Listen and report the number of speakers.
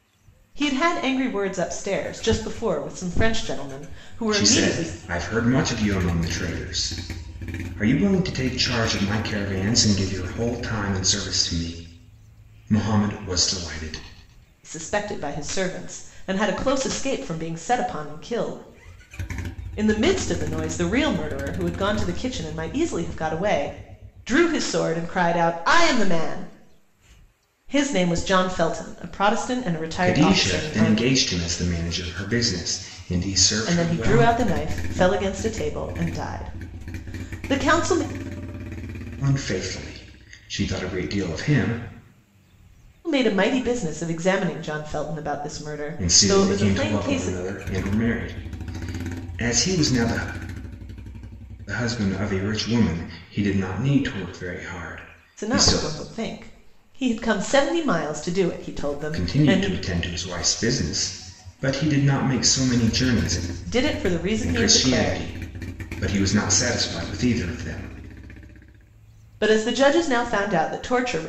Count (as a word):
two